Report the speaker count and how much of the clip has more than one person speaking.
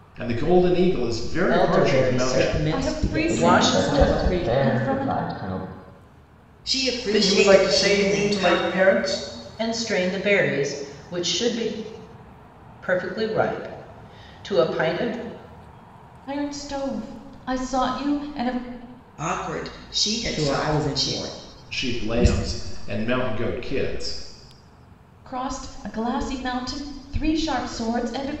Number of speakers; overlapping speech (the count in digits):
7, about 24%